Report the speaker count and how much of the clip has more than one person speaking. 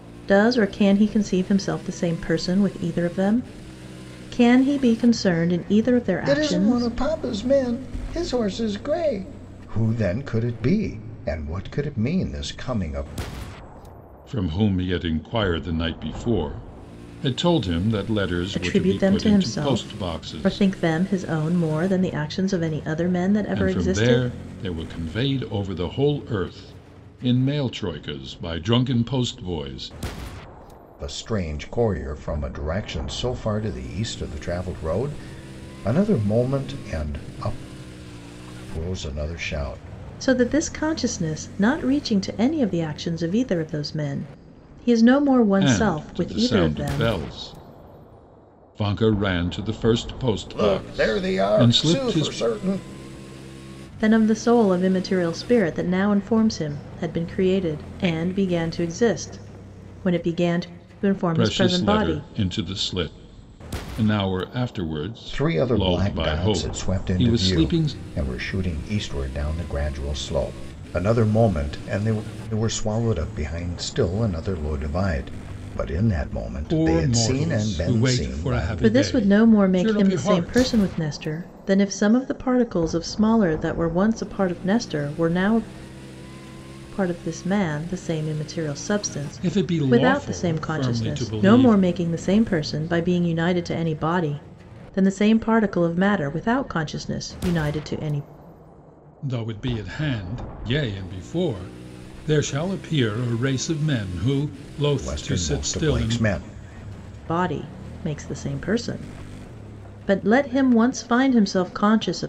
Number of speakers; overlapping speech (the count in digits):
3, about 17%